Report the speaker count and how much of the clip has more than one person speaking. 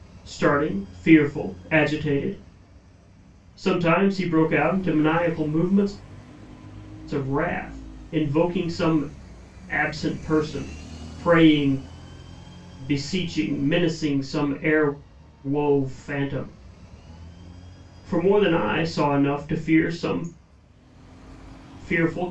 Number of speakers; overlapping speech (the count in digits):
1, no overlap